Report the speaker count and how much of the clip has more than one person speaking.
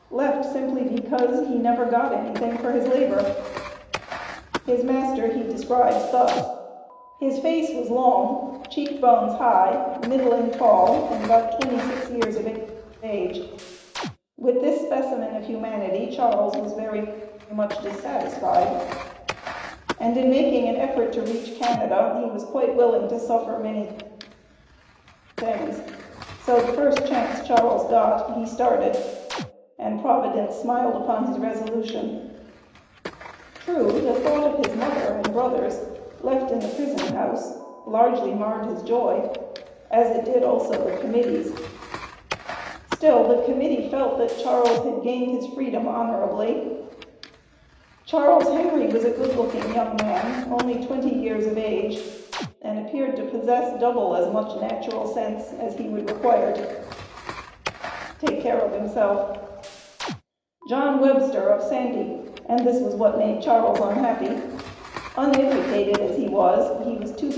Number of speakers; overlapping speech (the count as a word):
one, no overlap